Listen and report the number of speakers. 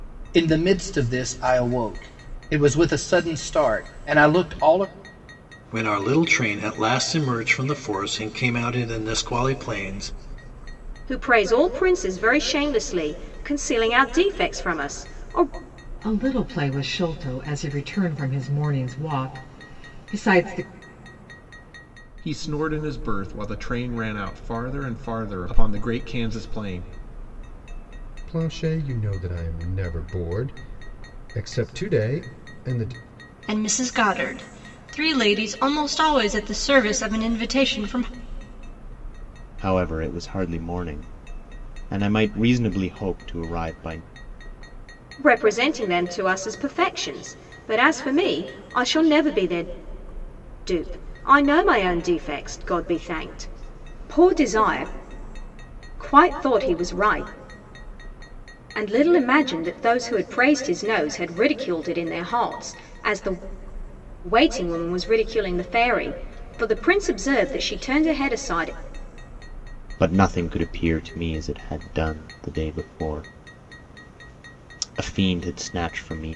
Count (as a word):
eight